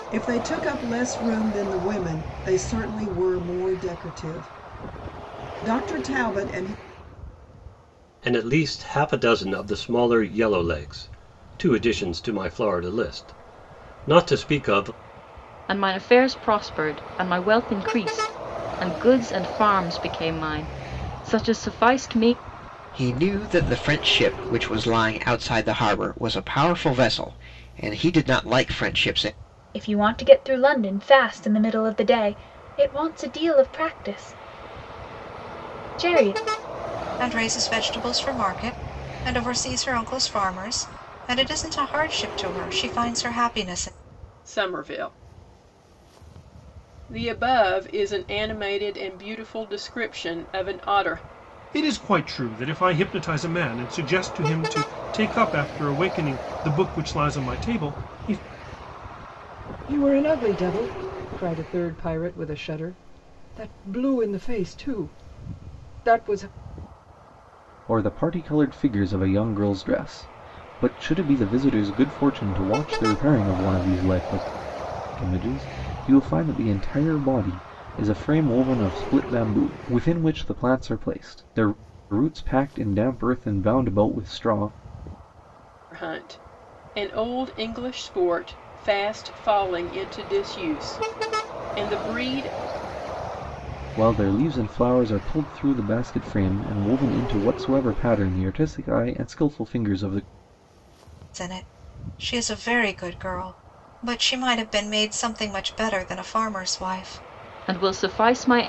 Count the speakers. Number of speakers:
10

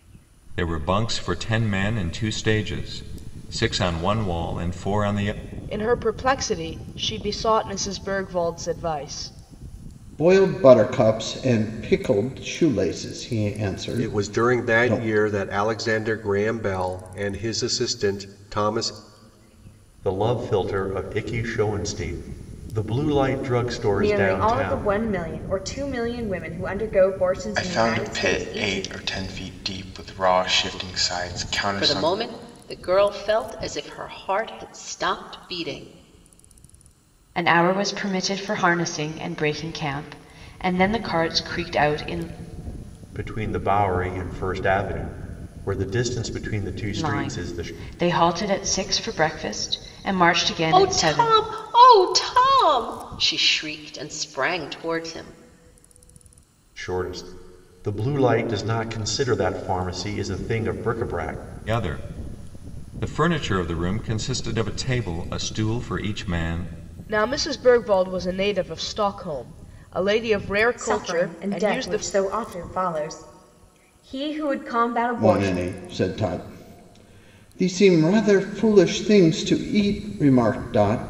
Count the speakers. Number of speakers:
9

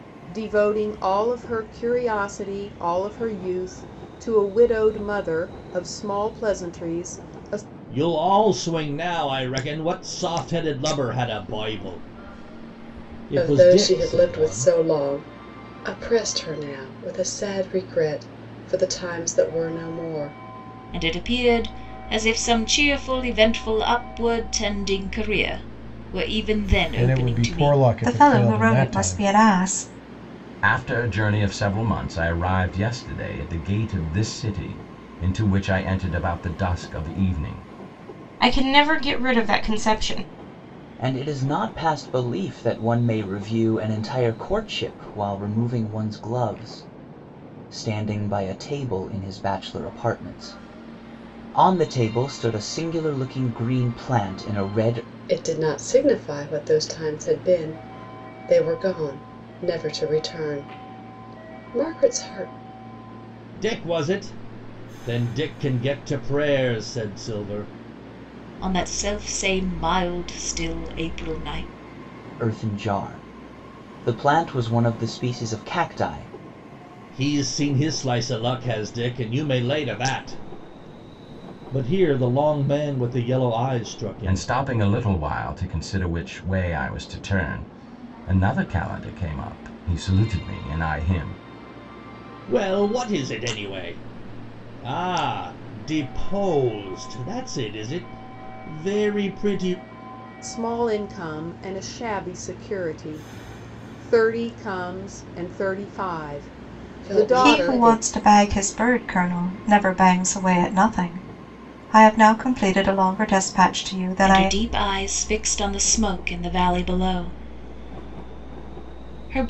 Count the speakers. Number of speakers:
9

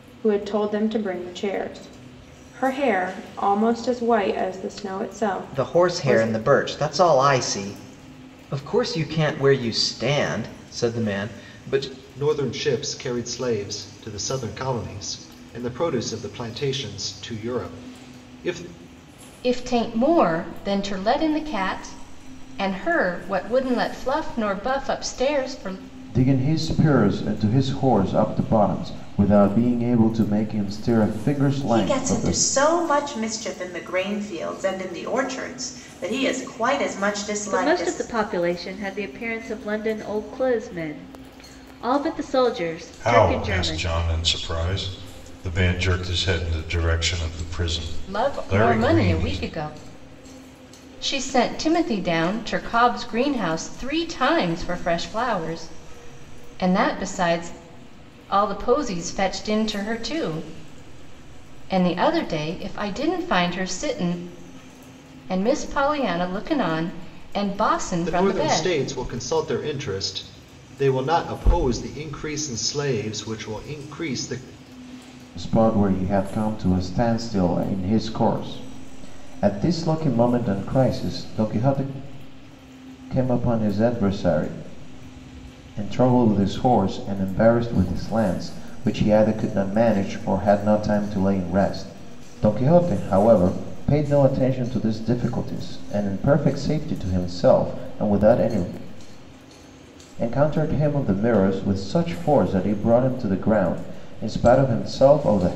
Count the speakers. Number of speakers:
8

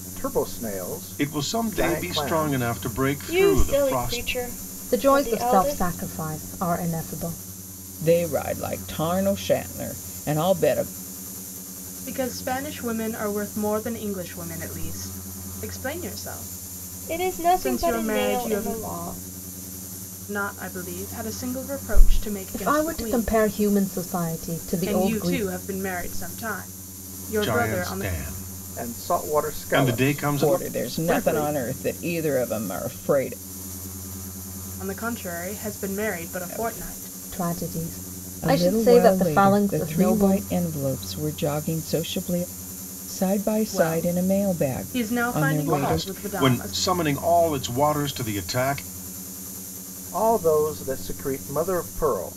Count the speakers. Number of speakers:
6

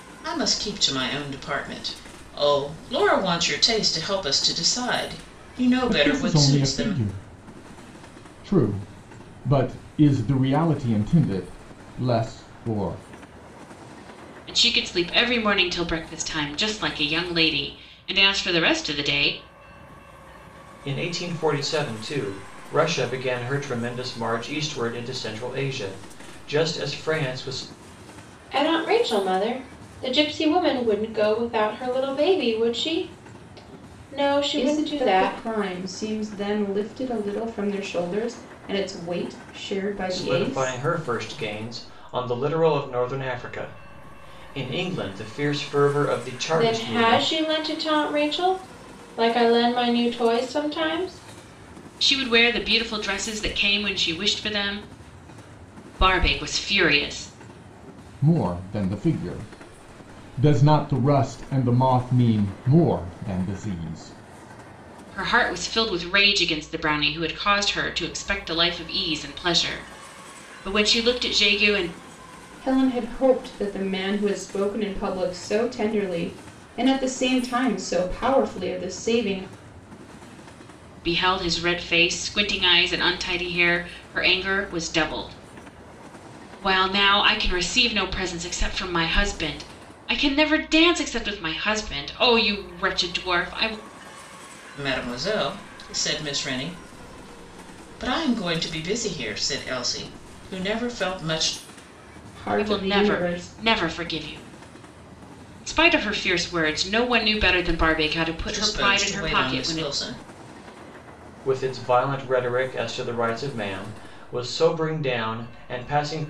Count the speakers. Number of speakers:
6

